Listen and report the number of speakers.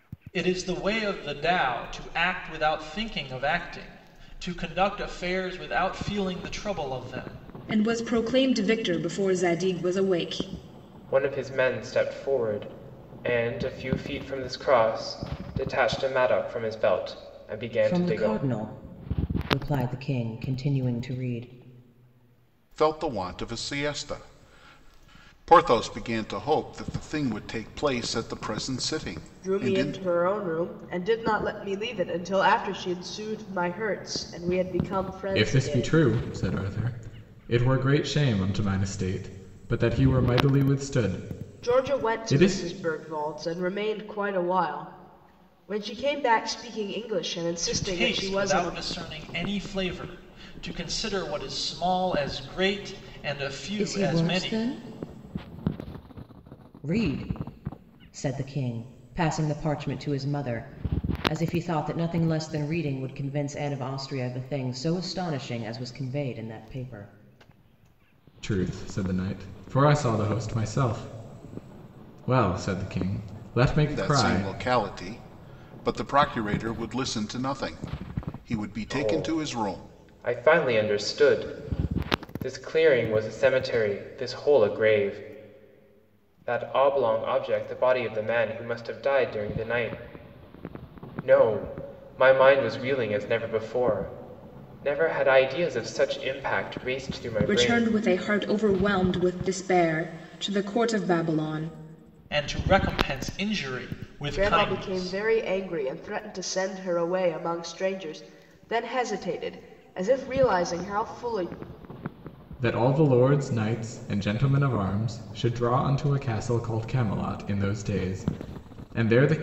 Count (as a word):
seven